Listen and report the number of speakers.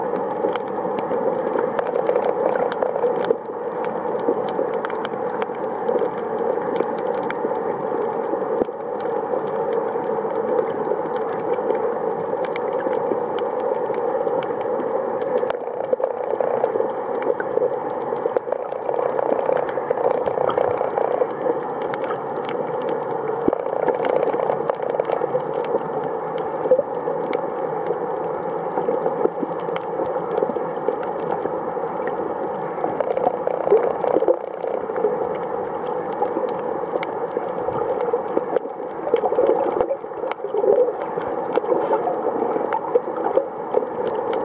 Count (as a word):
zero